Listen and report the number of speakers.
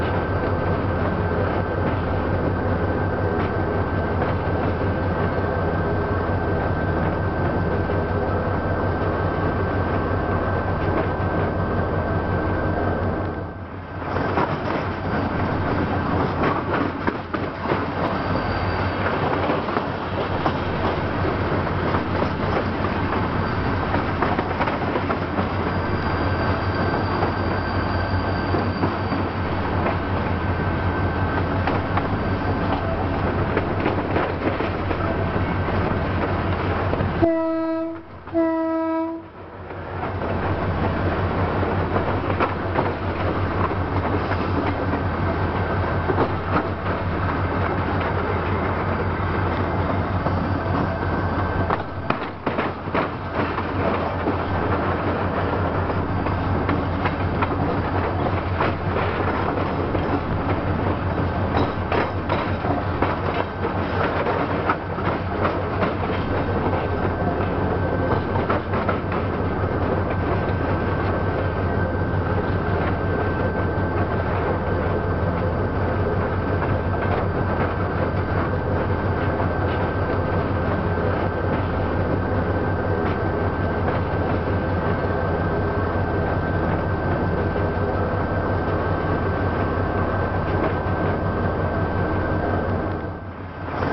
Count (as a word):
zero